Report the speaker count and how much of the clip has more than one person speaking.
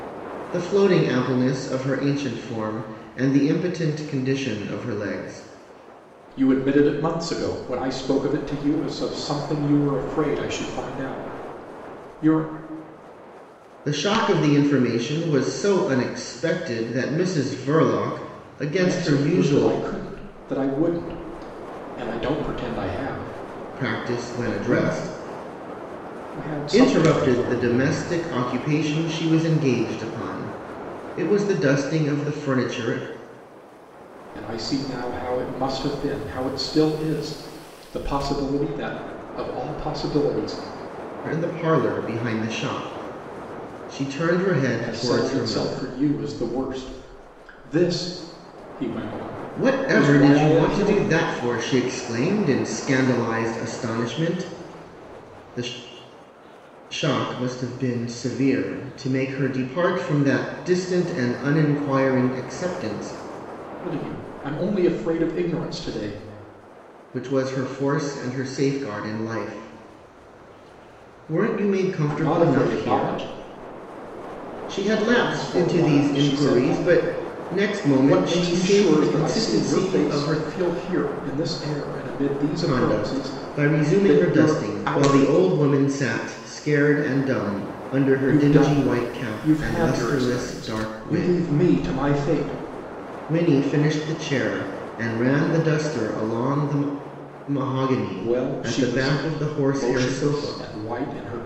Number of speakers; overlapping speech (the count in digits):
2, about 21%